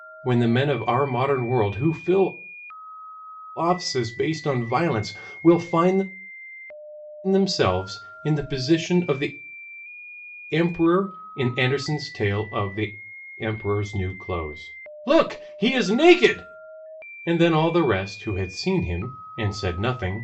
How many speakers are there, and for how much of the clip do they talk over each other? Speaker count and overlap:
1, no overlap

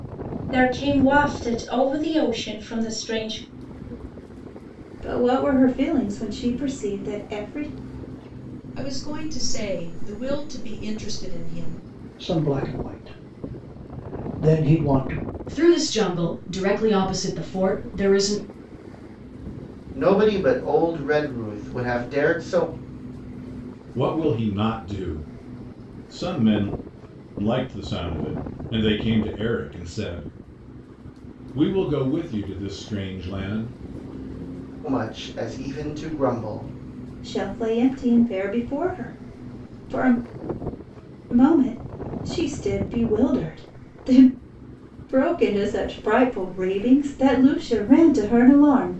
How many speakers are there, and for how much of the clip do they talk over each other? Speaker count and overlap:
7, no overlap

